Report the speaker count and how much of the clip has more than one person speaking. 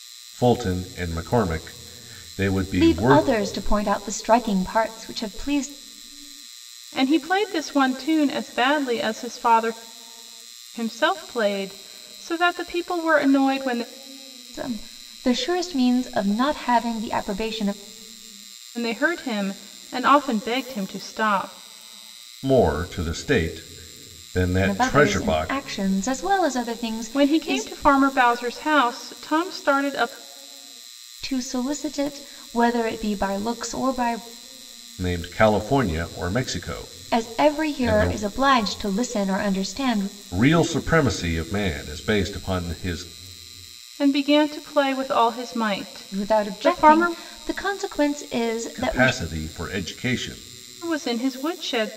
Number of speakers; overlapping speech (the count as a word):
three, about 9%